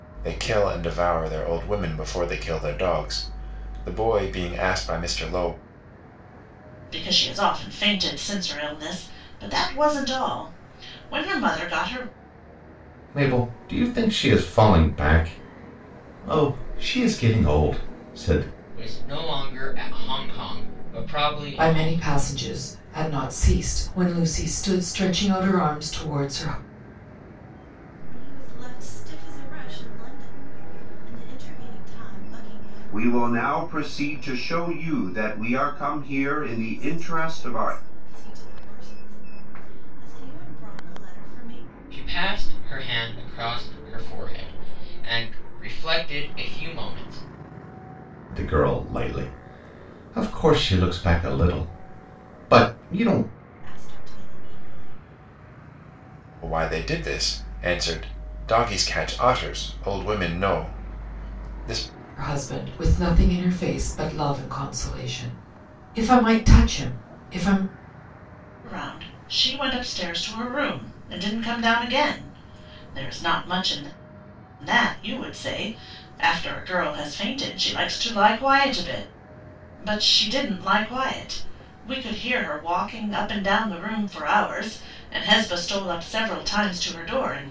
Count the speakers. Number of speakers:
7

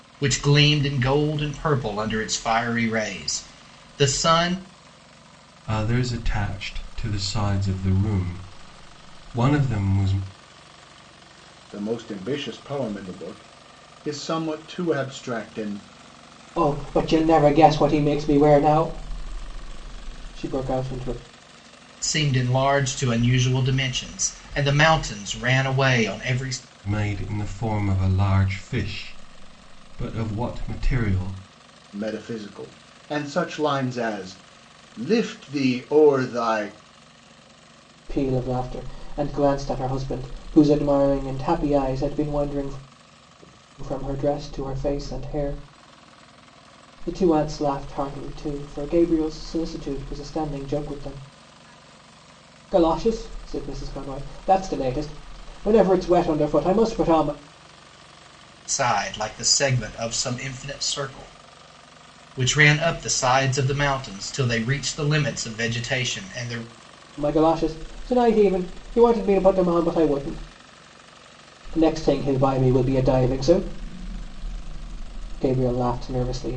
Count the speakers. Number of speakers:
4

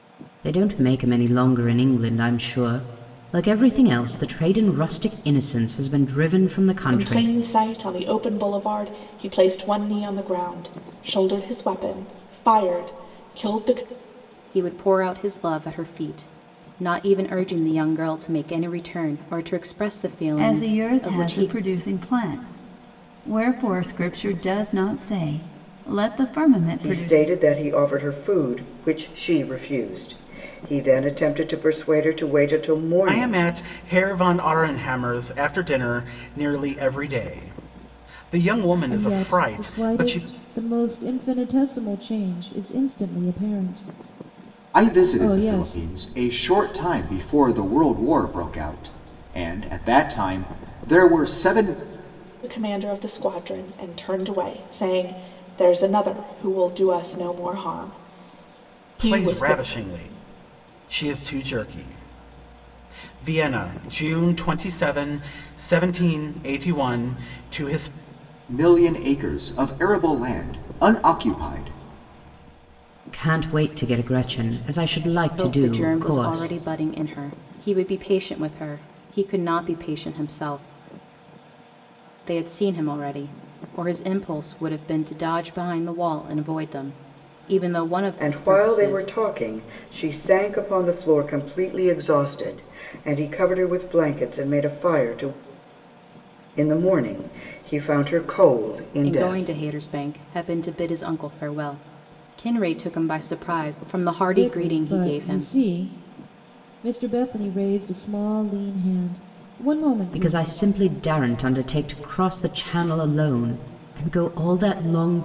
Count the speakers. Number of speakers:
8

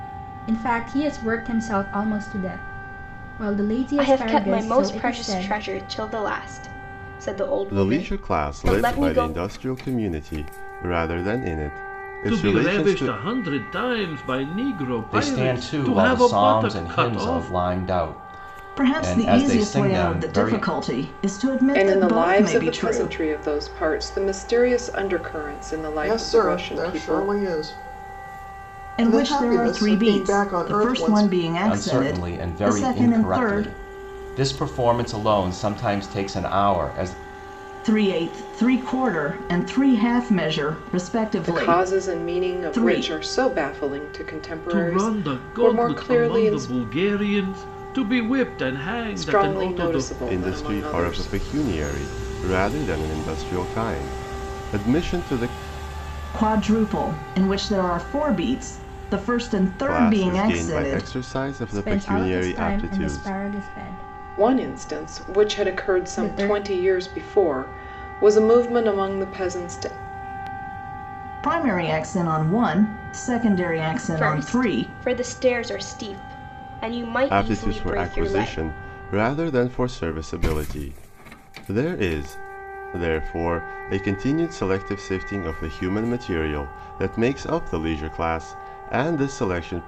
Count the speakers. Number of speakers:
8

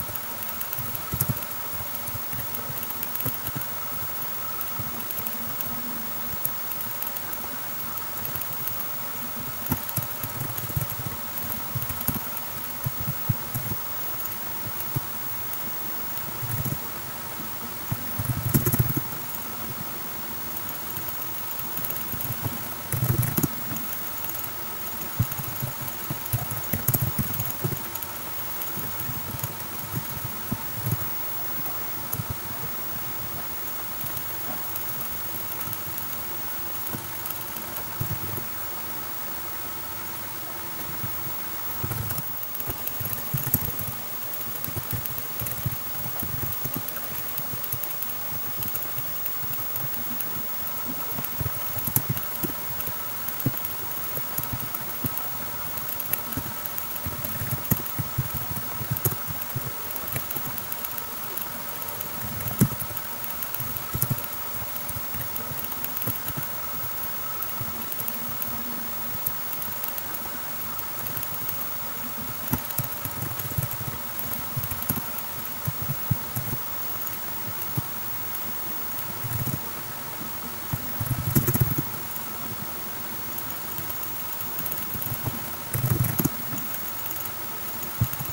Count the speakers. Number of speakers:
0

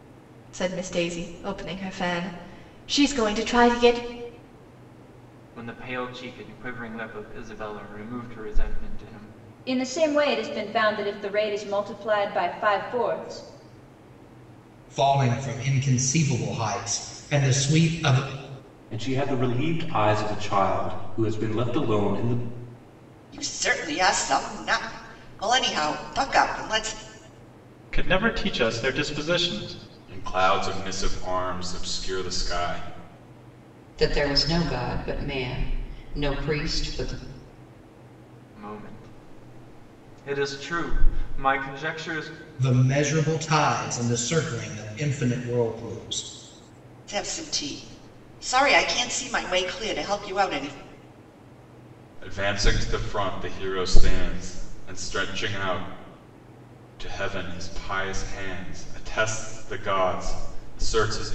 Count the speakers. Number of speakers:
9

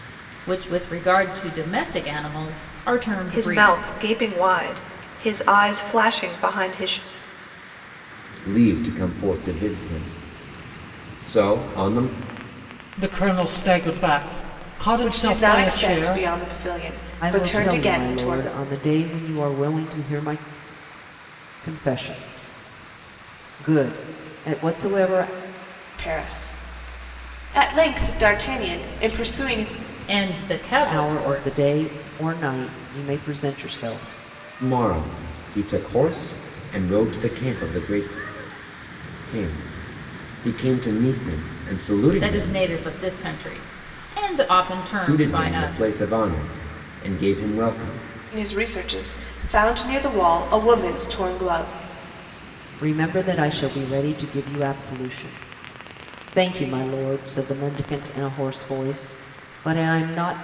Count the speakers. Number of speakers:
6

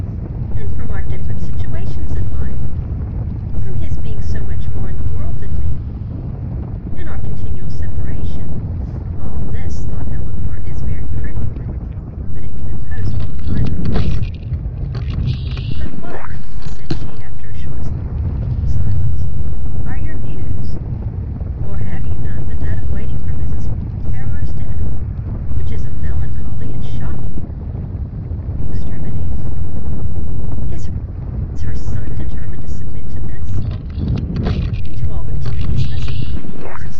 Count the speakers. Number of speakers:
1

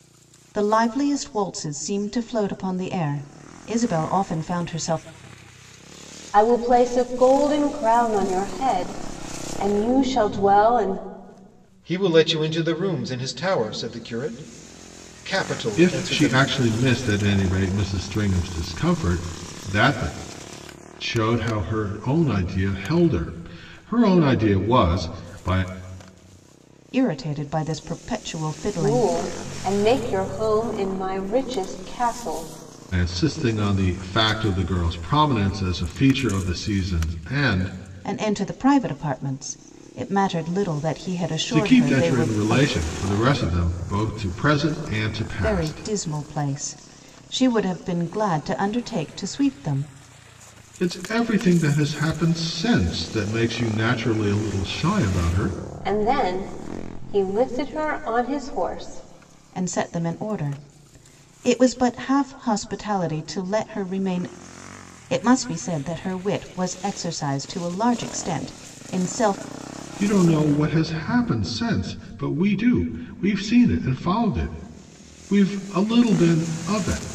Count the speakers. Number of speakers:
4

